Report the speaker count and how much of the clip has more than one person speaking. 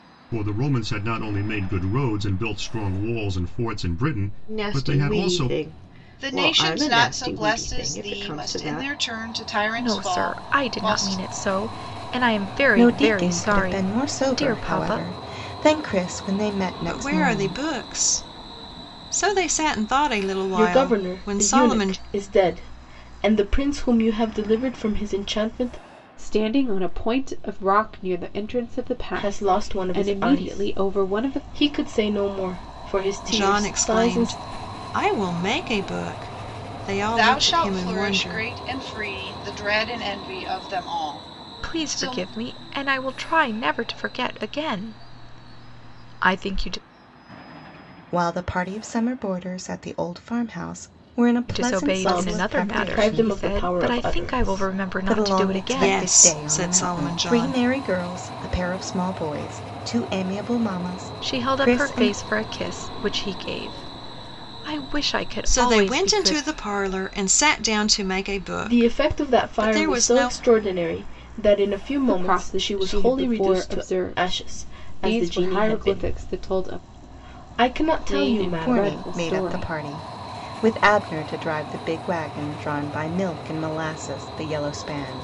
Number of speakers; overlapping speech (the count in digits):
8, about 37%